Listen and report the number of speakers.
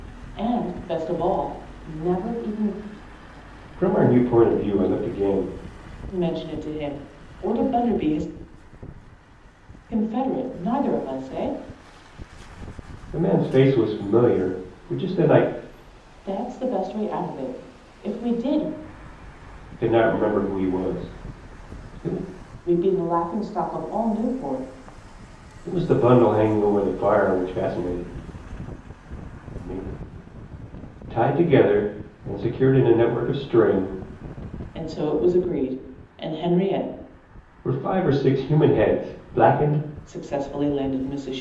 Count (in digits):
2